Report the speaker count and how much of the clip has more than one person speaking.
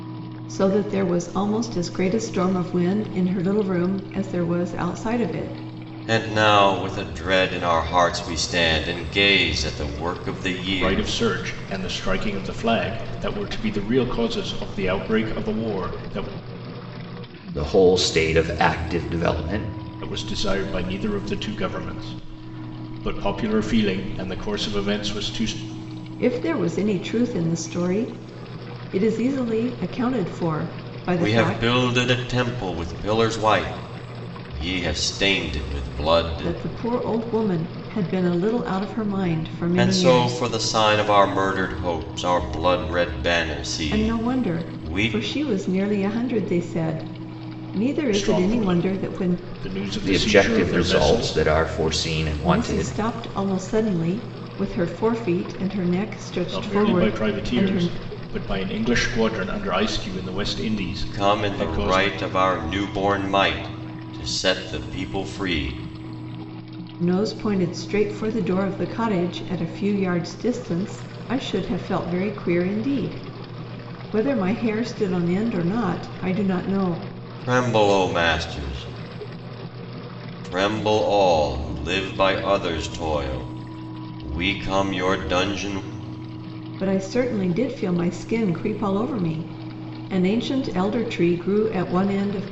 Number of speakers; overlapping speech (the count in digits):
4, about 10%